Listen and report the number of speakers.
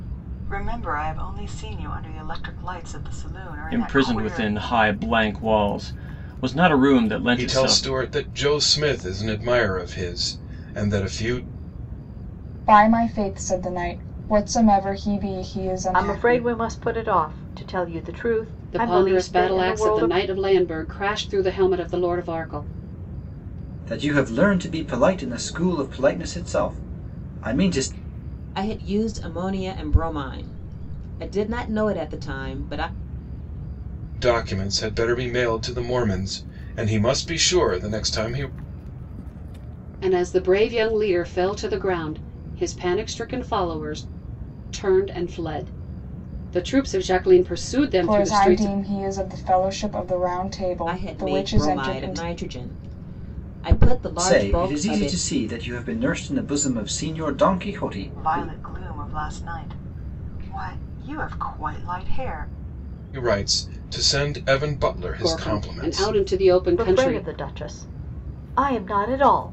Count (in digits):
8